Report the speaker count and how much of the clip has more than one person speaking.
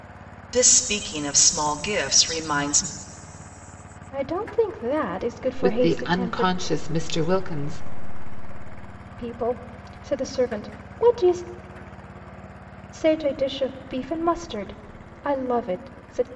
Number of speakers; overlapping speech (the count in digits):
3, about 6%